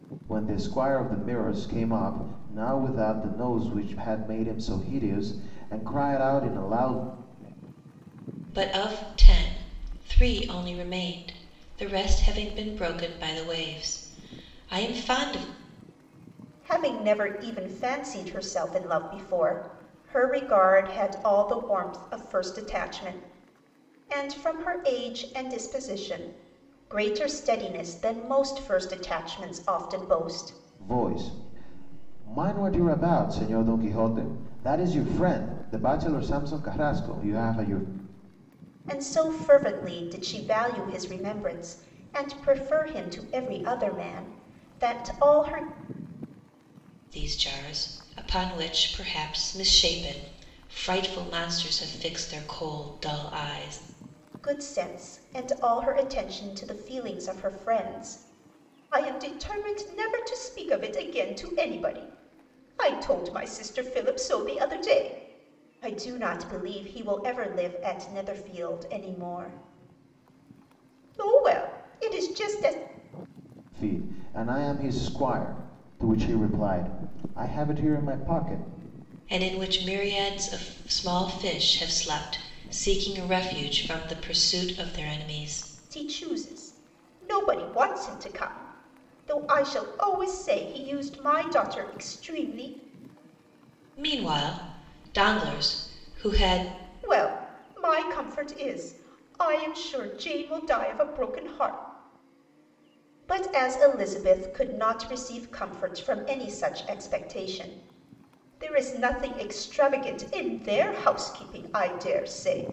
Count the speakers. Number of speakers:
three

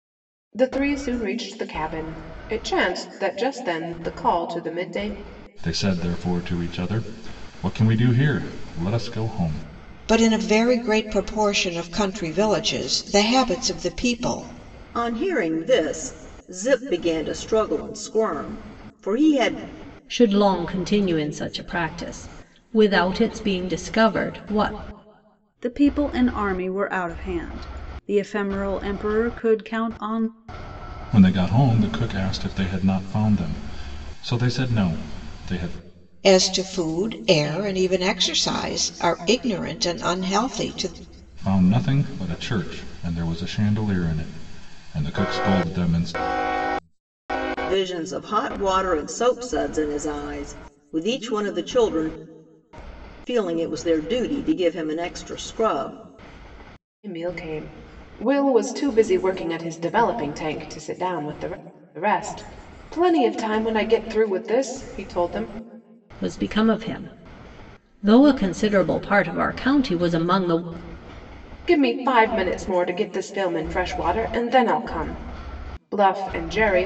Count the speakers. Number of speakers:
six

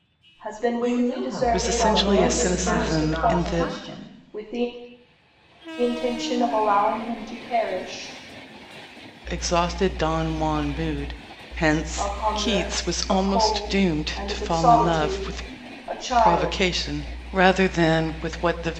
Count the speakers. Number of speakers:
four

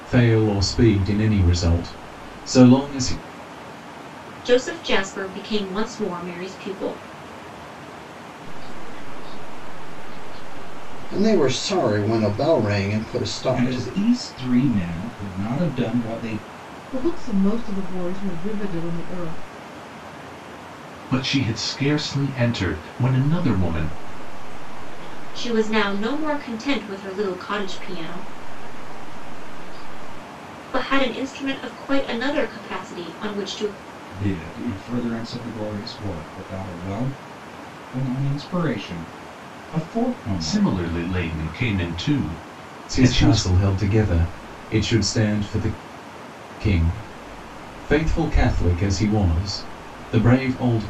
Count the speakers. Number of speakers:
seven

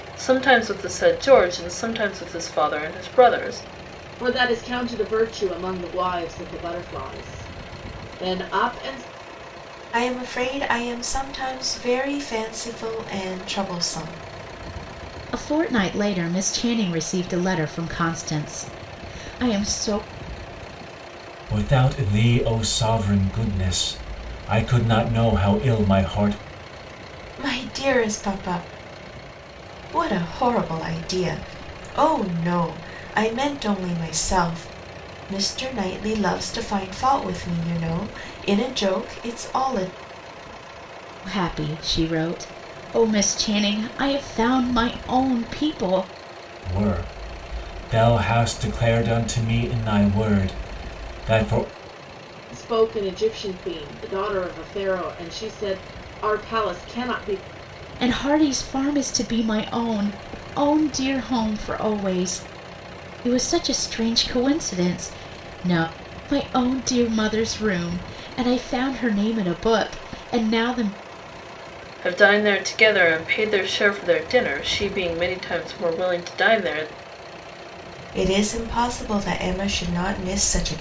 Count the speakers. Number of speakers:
five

